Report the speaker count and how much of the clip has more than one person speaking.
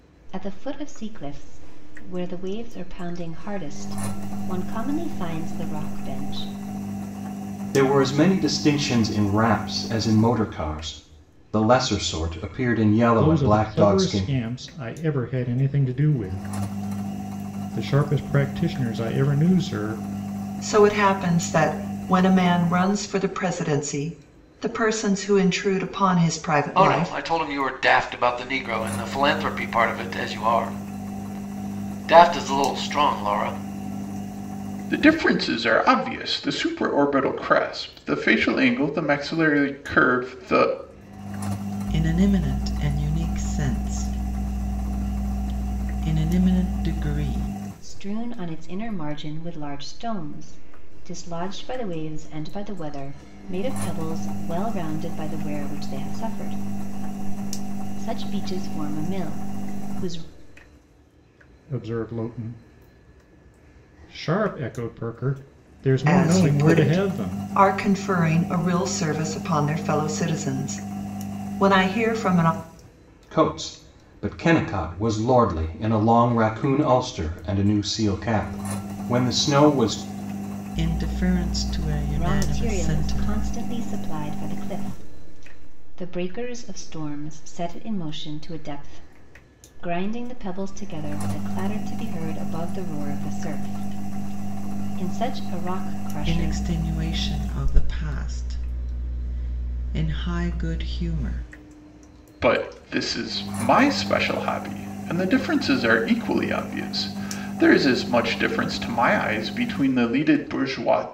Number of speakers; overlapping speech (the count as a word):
seven, about 4%